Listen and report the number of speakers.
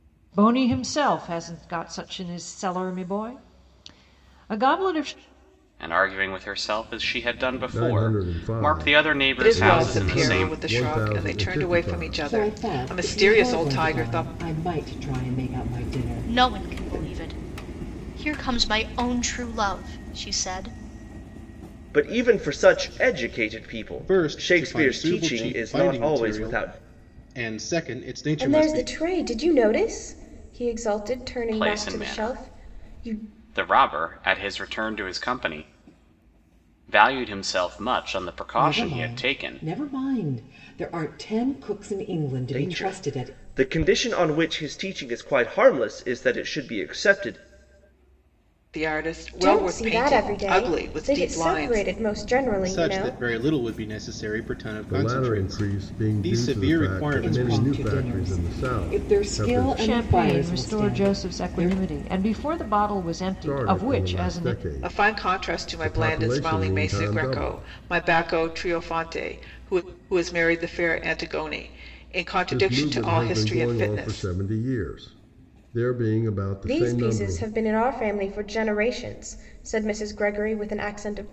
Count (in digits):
9